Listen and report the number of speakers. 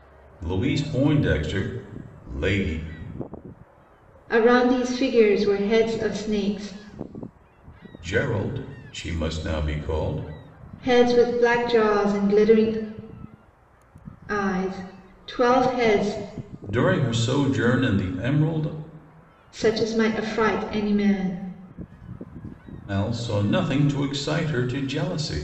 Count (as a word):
two